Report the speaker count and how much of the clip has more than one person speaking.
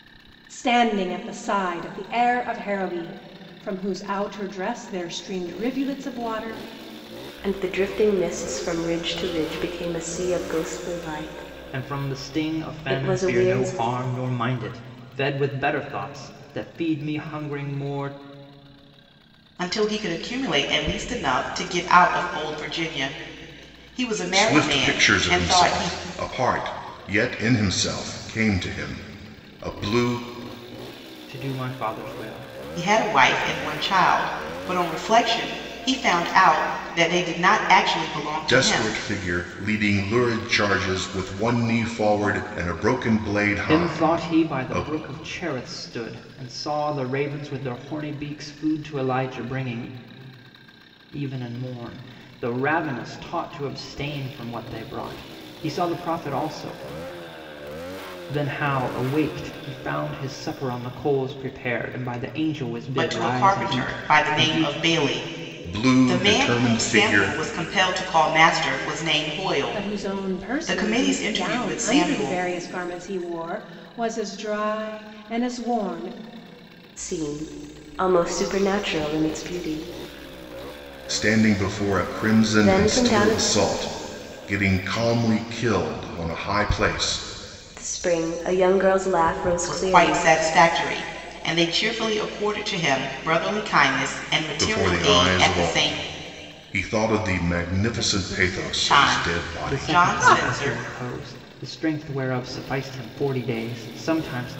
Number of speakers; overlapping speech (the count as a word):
five, about 18%